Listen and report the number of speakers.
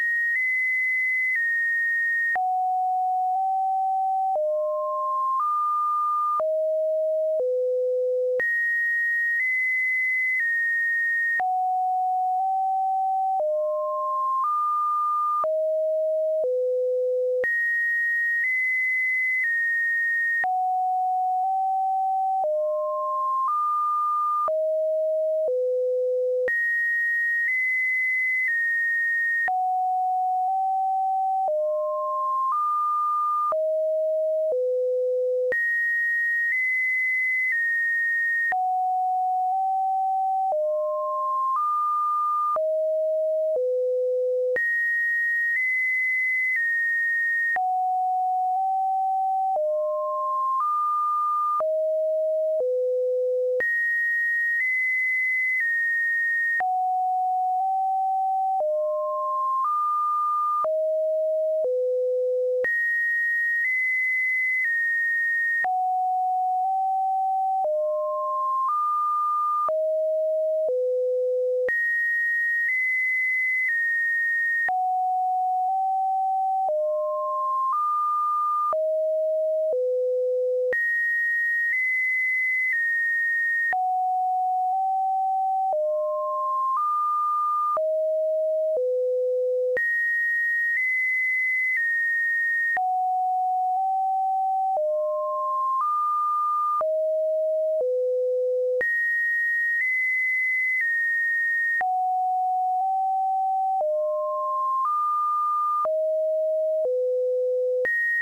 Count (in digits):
0